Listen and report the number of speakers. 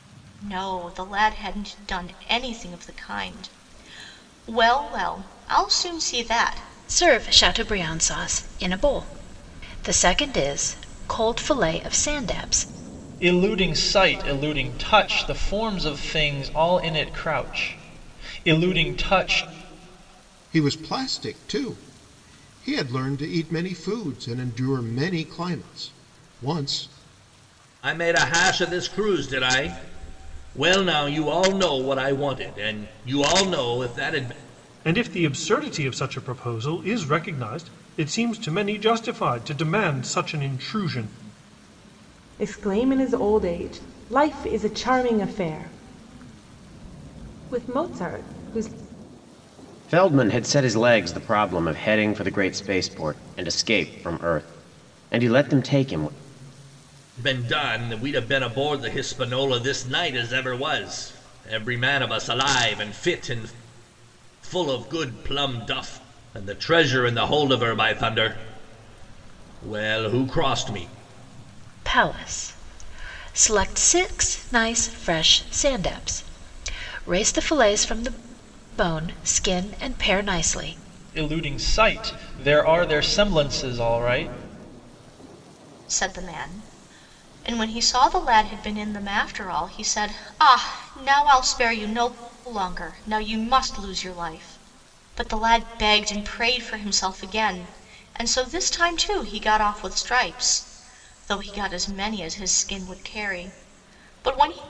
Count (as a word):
eight